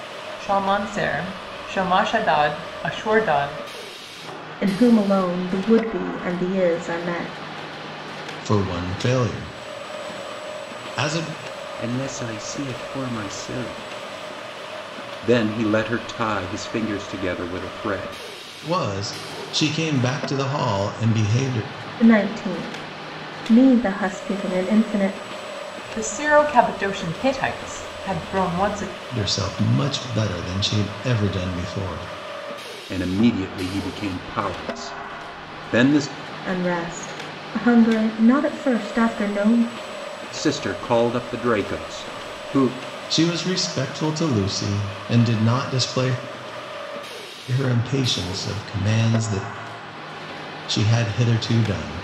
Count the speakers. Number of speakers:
four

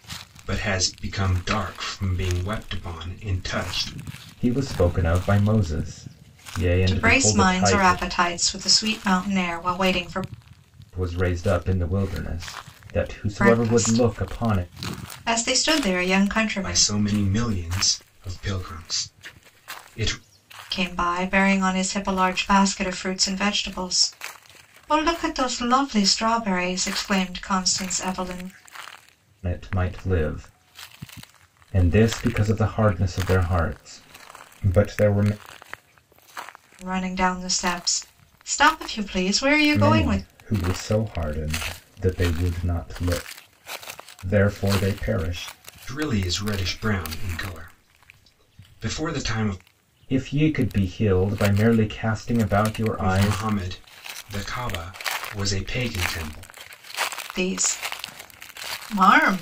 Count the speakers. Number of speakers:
three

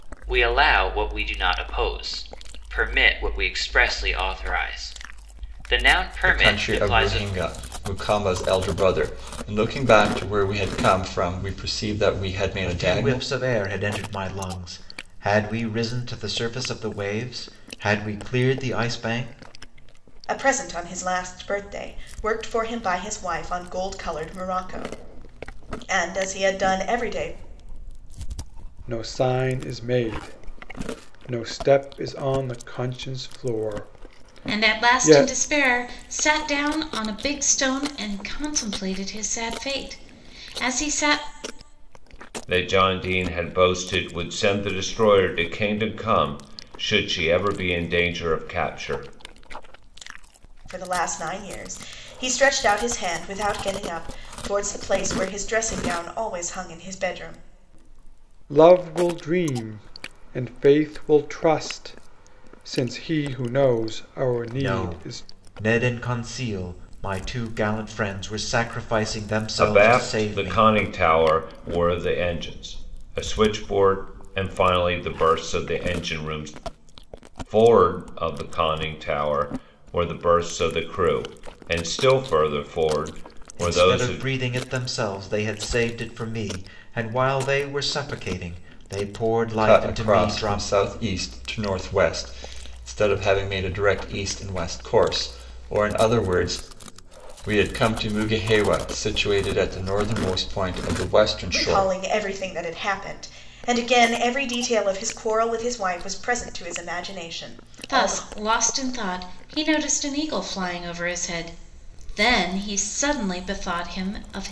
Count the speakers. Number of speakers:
seven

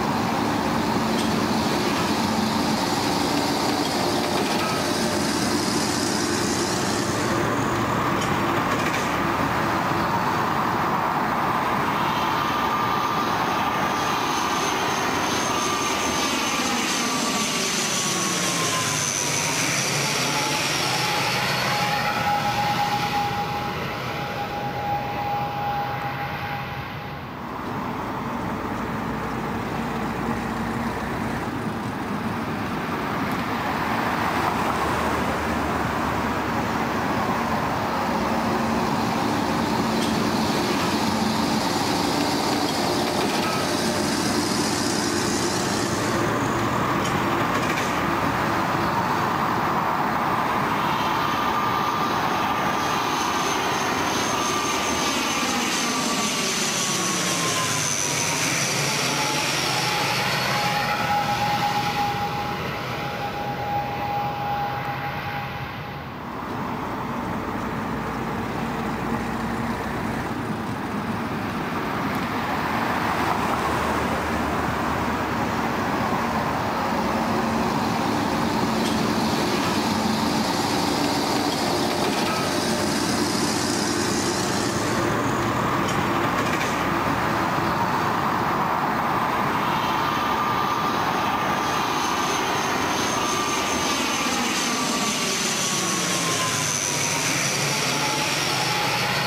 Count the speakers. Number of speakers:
zero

